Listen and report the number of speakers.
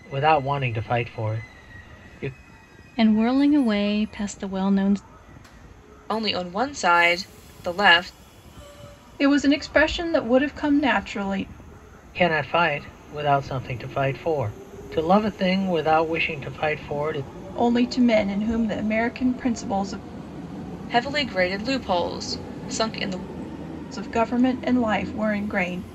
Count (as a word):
four